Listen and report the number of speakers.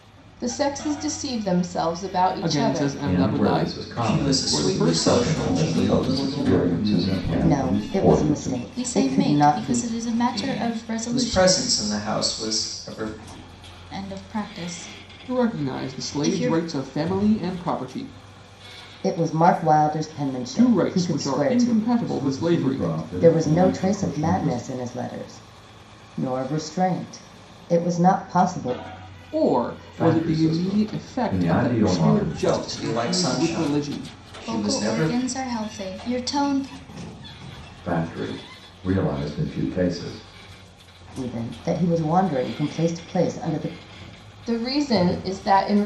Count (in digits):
8